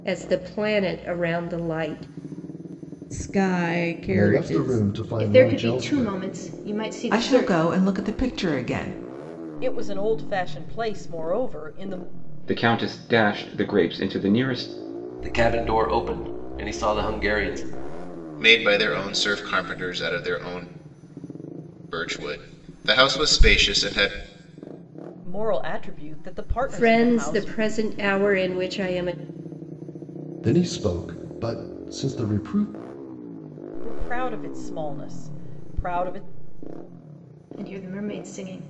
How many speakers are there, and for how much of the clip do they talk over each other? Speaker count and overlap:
9, about 8%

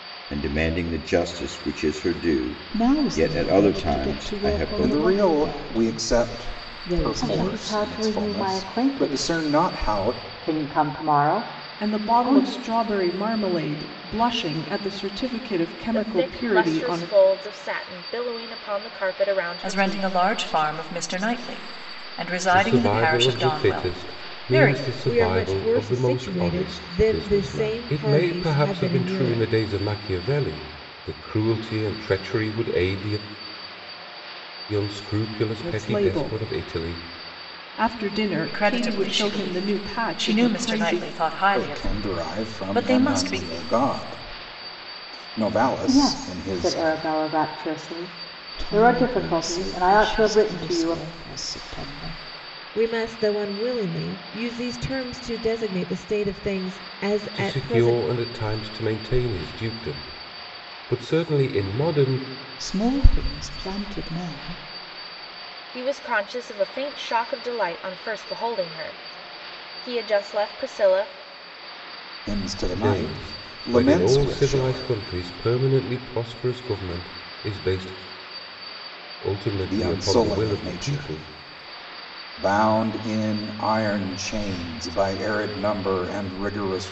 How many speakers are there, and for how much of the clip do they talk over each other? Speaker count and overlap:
9, about 35%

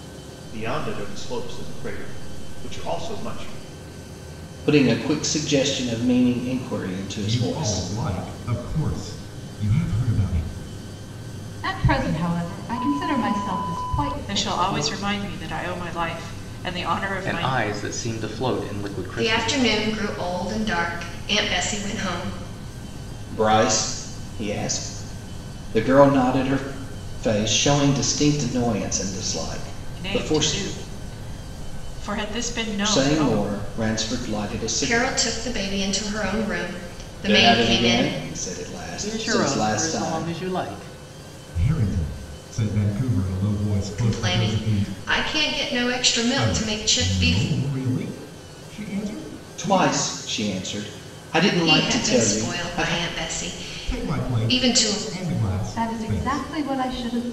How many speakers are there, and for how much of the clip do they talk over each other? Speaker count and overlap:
7, about 21%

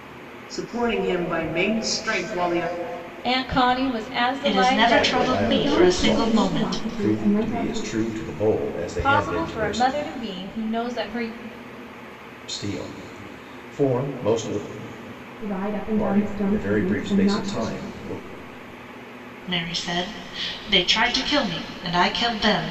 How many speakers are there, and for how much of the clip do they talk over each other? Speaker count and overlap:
5, about 27%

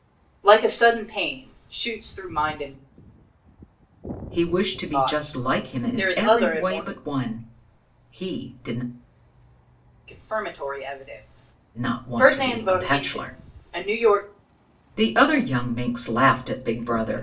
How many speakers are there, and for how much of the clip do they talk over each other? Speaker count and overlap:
2, about 20%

